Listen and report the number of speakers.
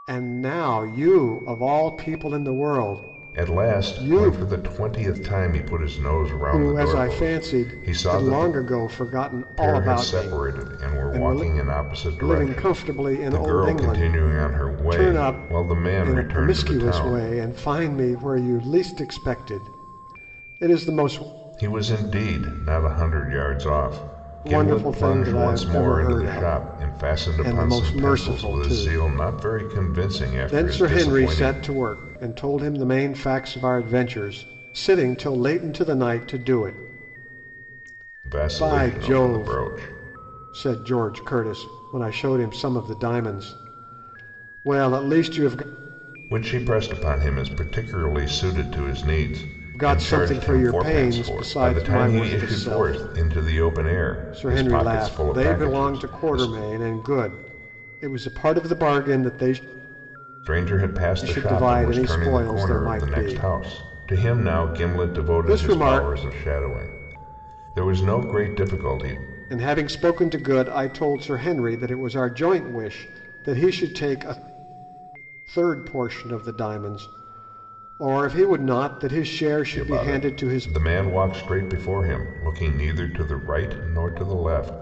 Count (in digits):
2